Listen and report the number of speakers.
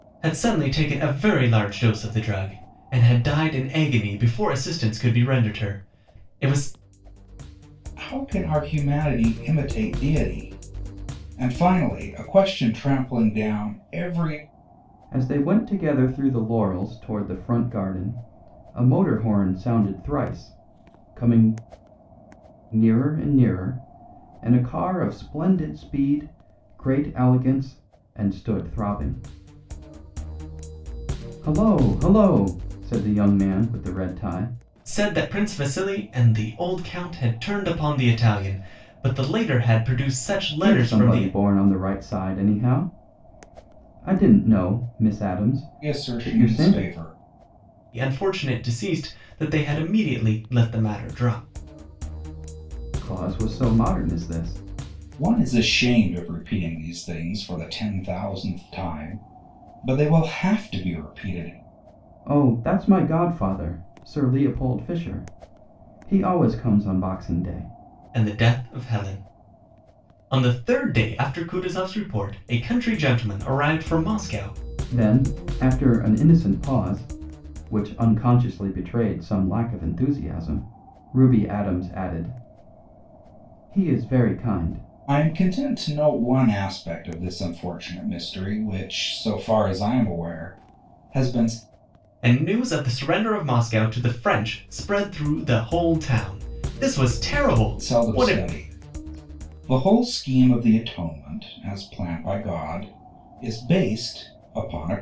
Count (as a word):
three